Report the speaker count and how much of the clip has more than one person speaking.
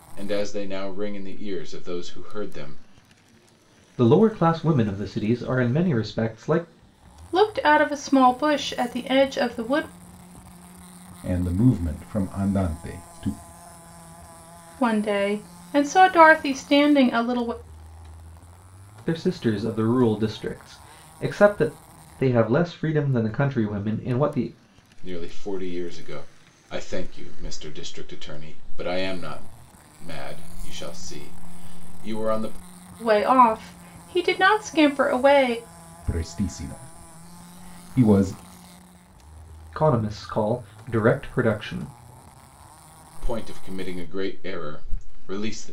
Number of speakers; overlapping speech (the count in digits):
4, no overlap